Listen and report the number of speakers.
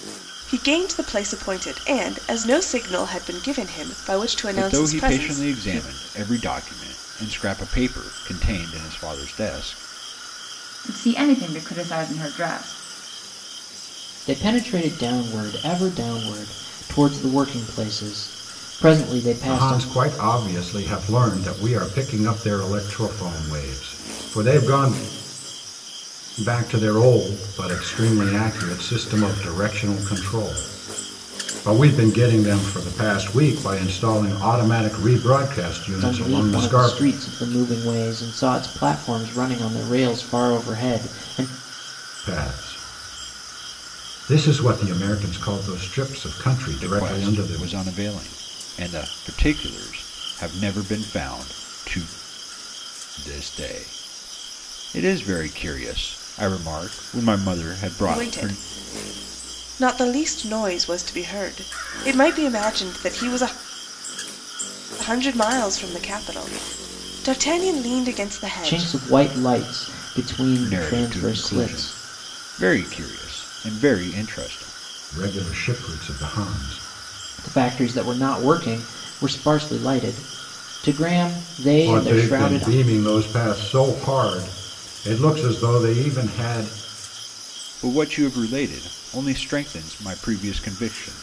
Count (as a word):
five